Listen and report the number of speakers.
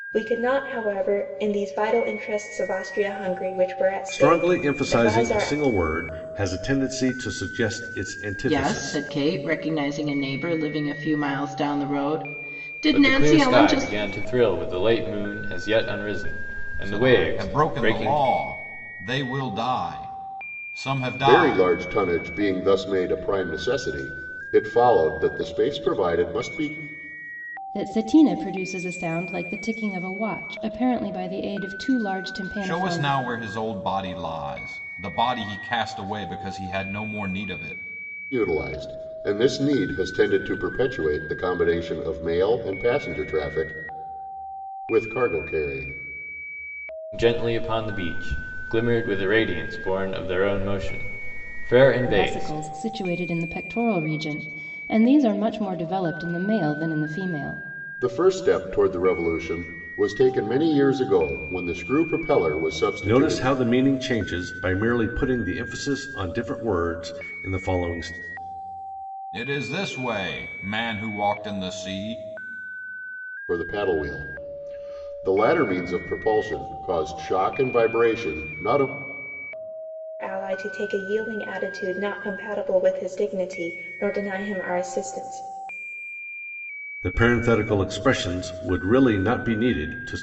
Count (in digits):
7